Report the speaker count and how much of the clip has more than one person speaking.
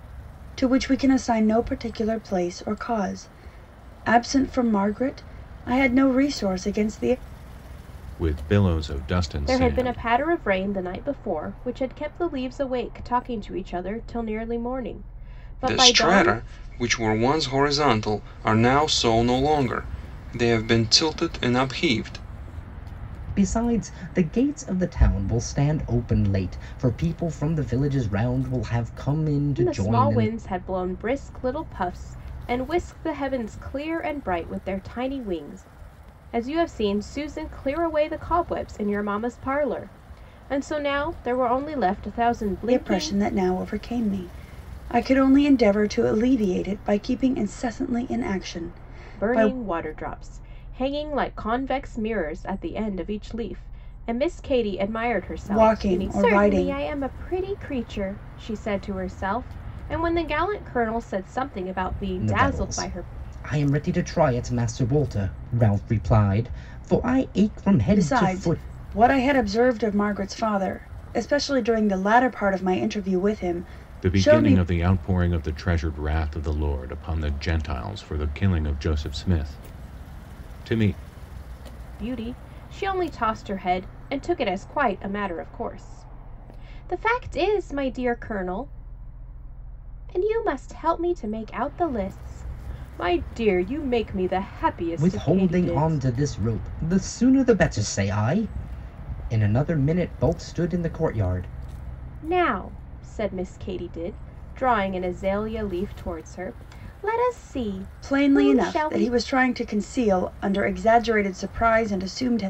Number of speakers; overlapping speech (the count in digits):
5, about 8%